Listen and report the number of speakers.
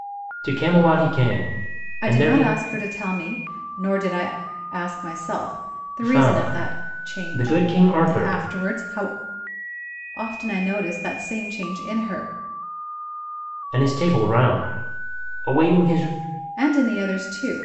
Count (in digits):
2